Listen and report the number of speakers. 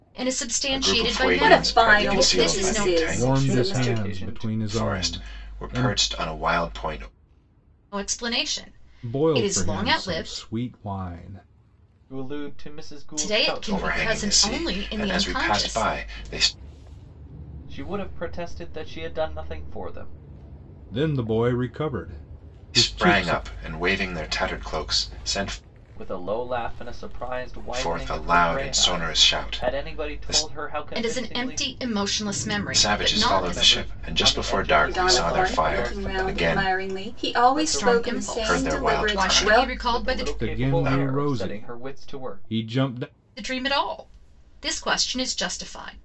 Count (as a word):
five